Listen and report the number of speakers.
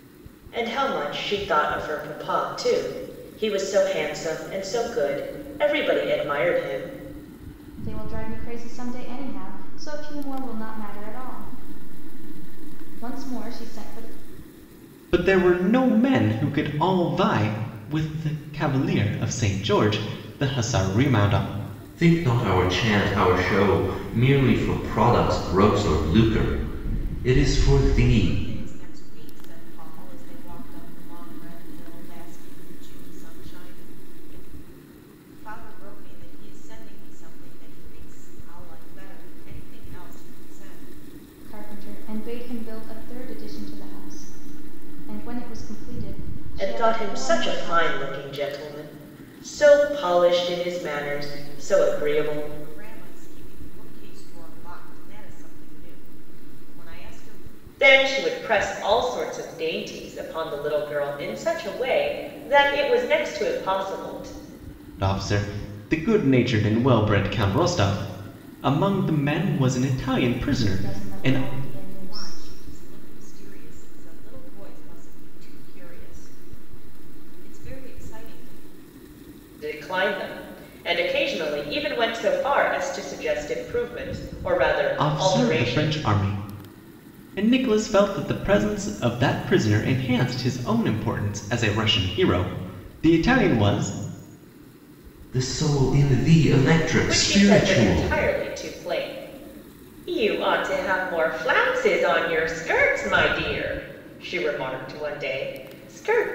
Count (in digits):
5